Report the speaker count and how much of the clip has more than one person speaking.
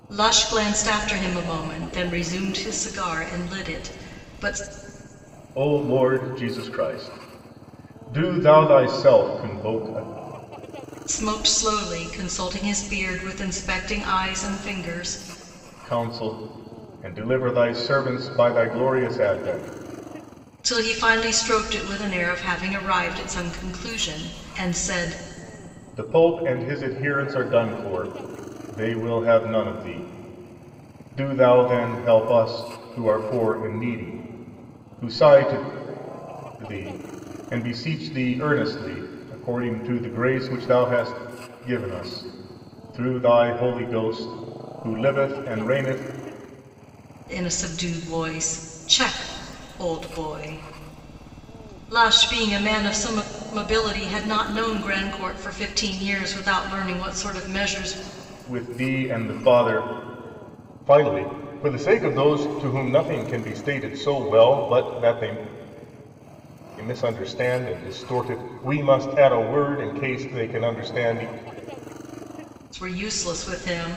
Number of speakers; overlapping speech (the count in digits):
2, no overlap